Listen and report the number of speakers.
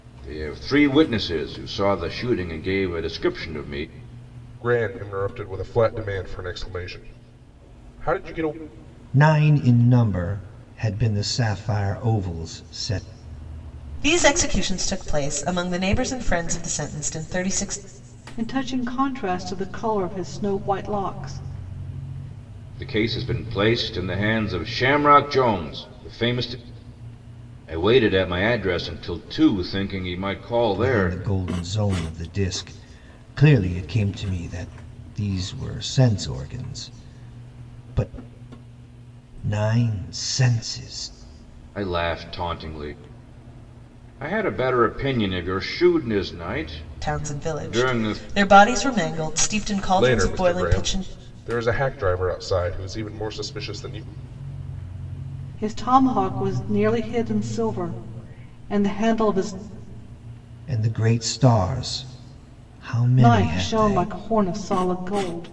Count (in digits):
5